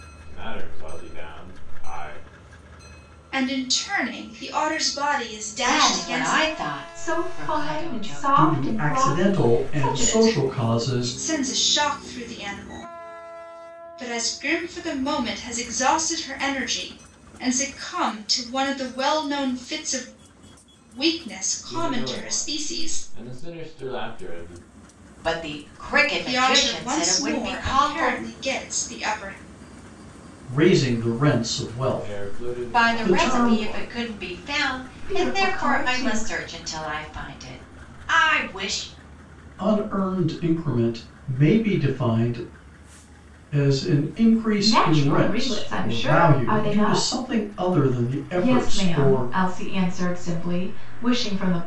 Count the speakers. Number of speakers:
5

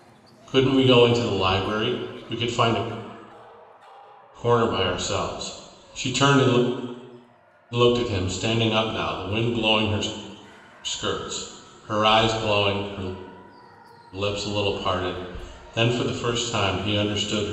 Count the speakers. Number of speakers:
1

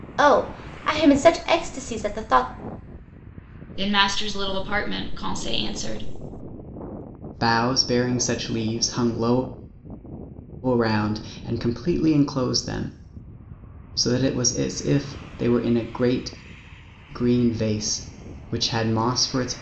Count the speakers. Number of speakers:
3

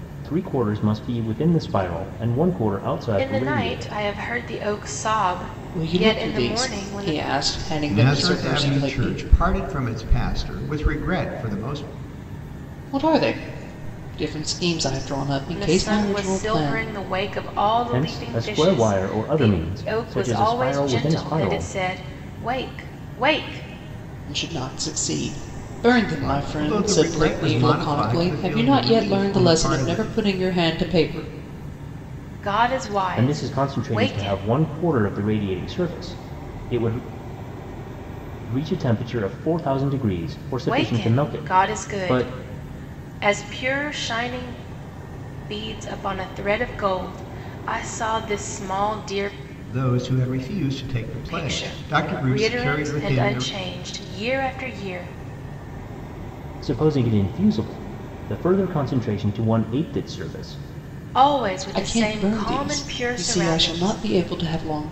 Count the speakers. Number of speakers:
4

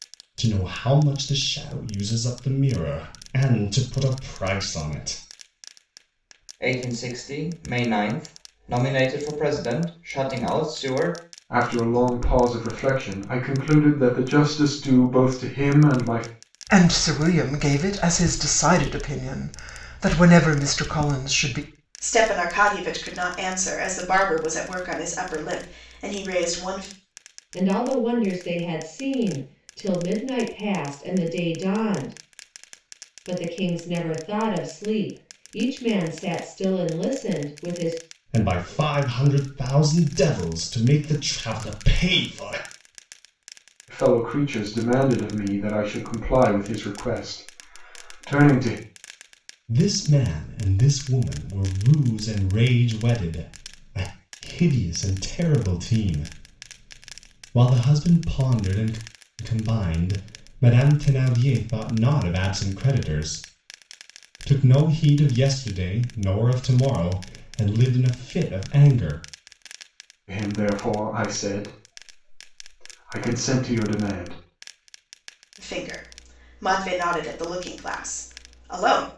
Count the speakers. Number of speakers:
6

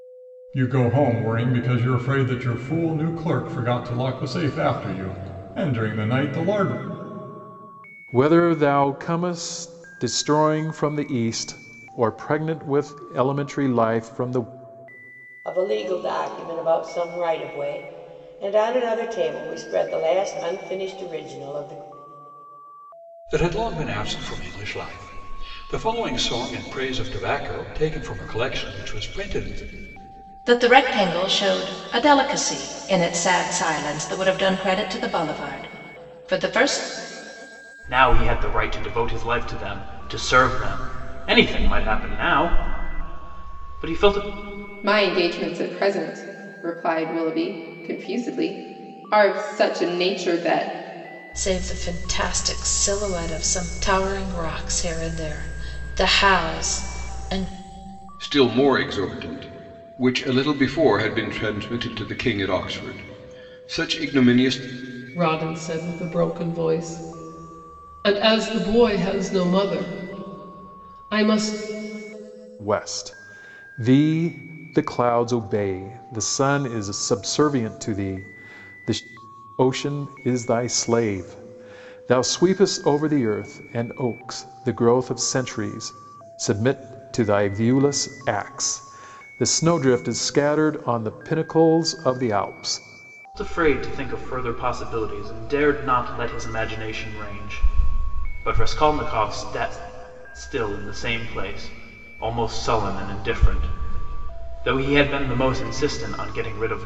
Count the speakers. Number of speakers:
10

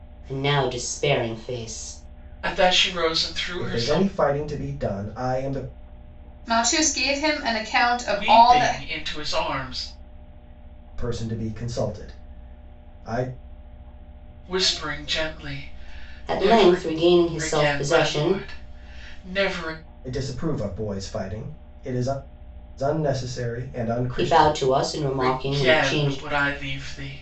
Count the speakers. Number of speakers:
4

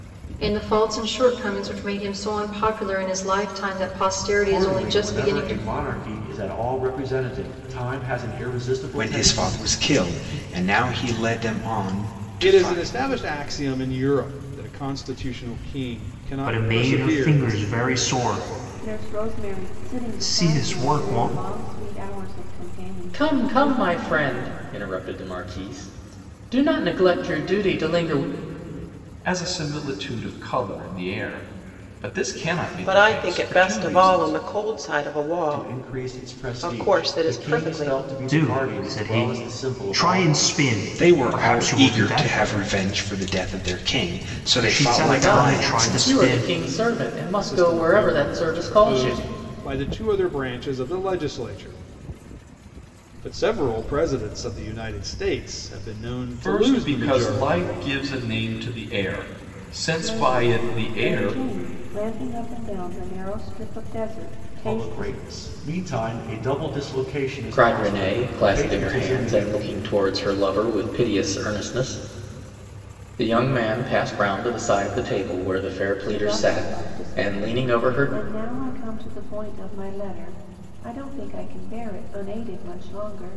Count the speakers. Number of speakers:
9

